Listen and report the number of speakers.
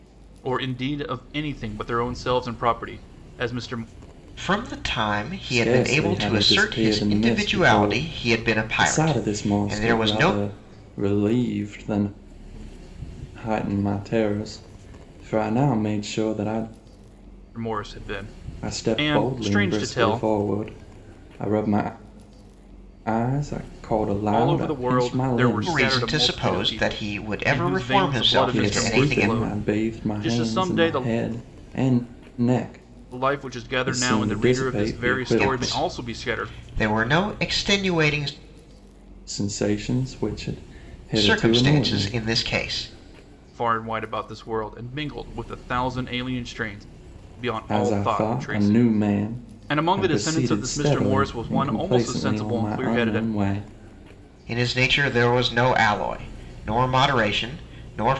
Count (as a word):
three